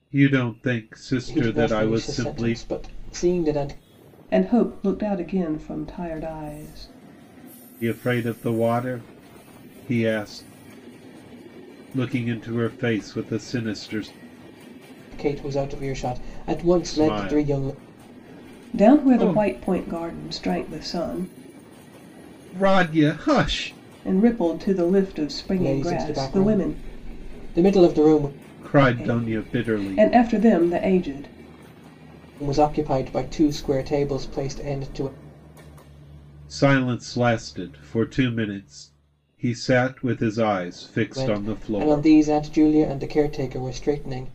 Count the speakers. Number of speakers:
three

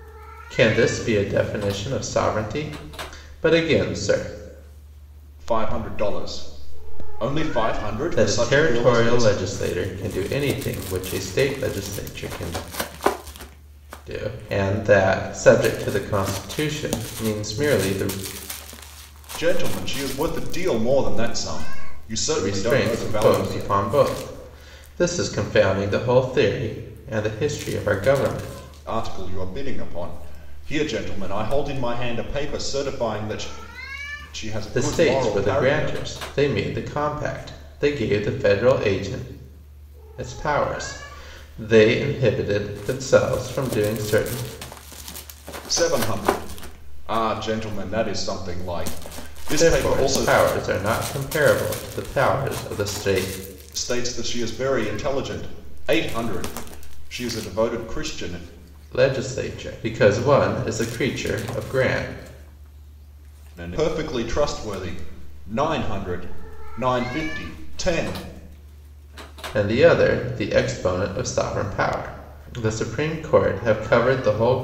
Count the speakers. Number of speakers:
two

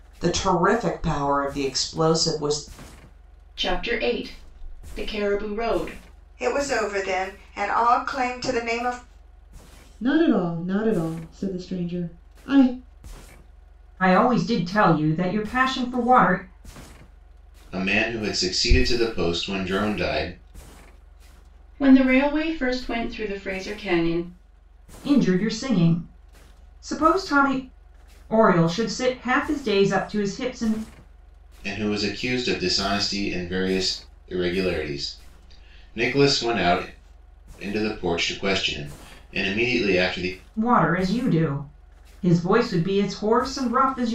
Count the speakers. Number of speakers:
six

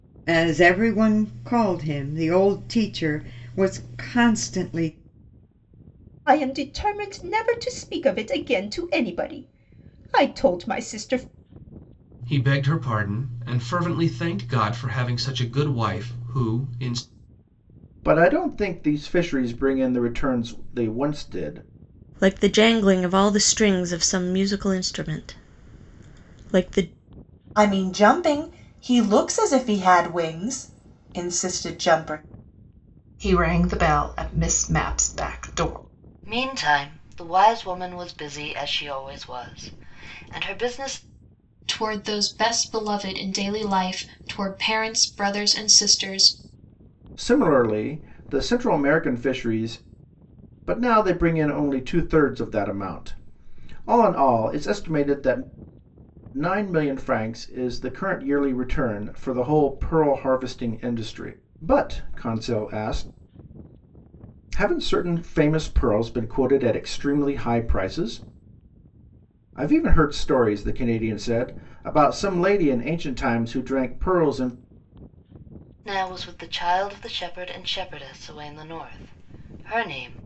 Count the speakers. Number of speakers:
nine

